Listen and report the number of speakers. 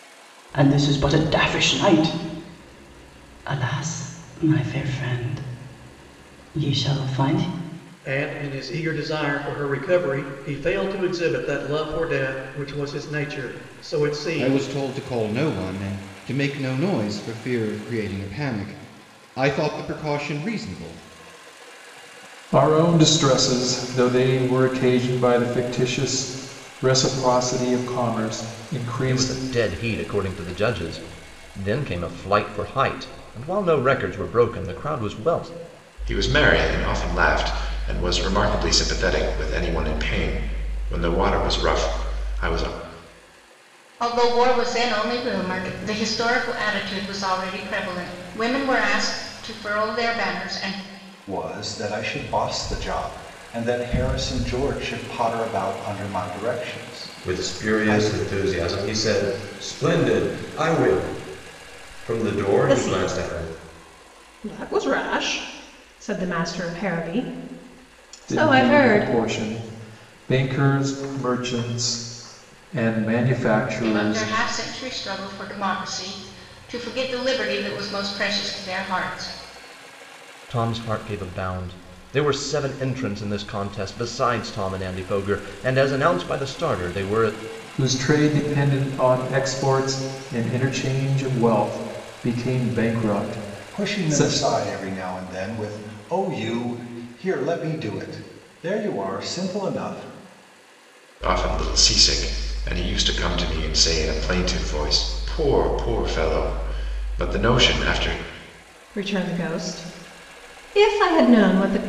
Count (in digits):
10